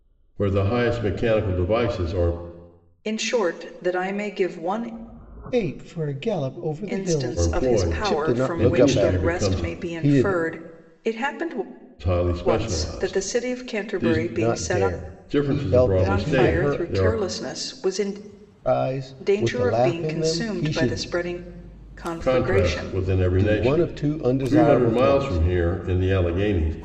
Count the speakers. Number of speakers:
3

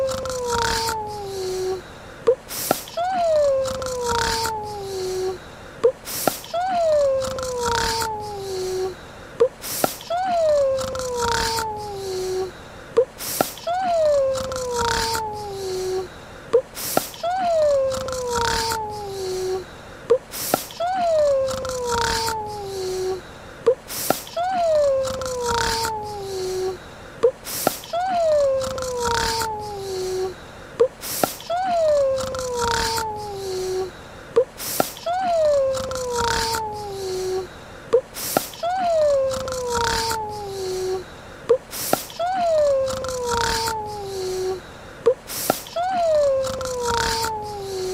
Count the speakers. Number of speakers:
0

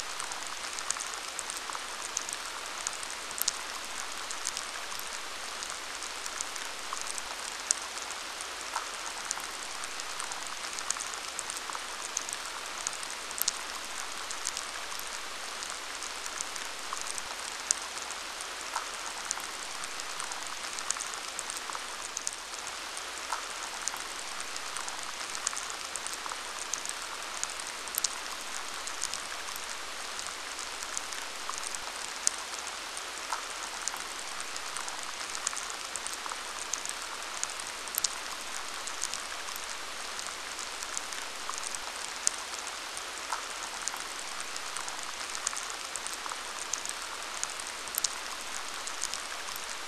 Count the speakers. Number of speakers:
0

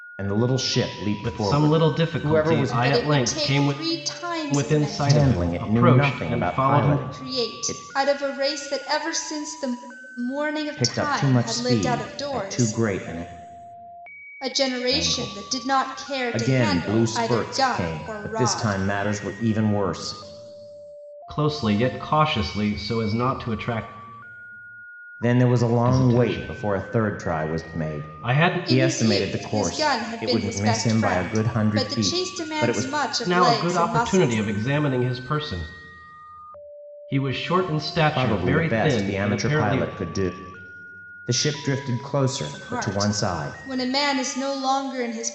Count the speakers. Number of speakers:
3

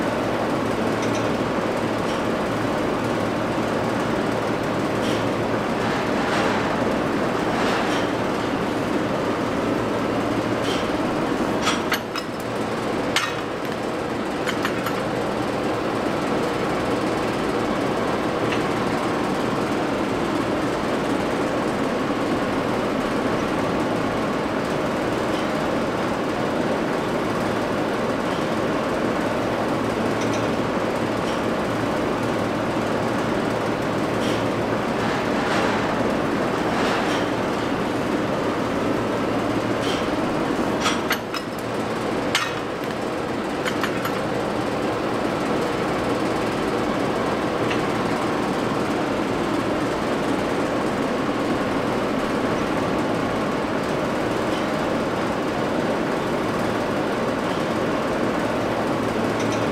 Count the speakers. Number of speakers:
0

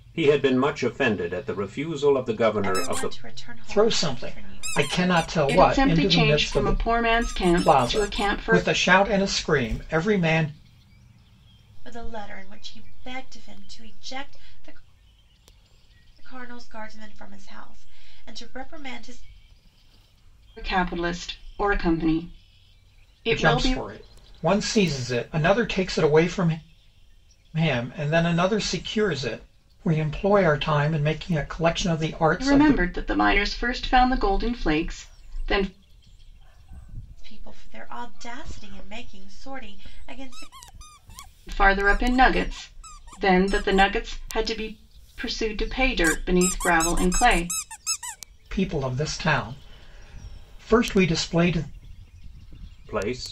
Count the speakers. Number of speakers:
4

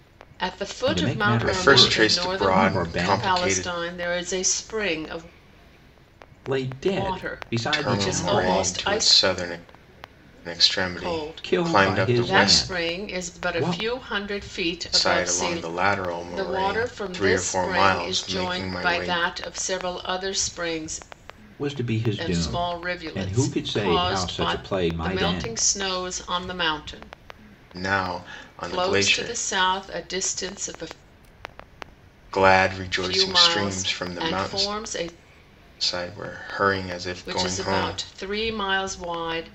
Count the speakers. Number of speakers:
3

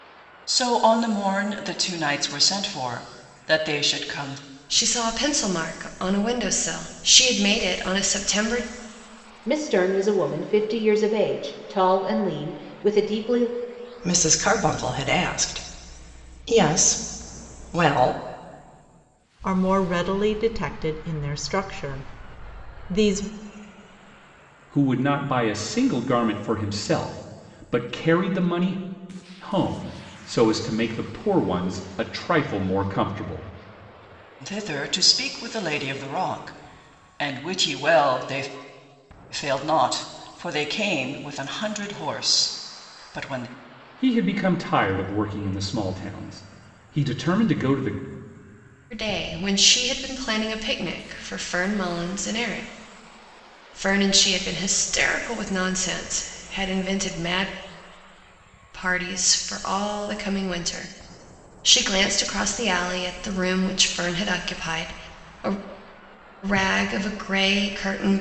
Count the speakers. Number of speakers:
6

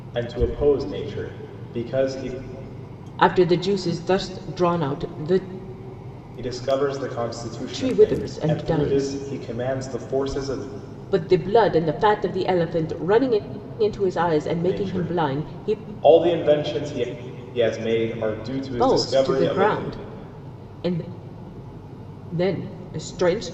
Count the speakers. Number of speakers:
2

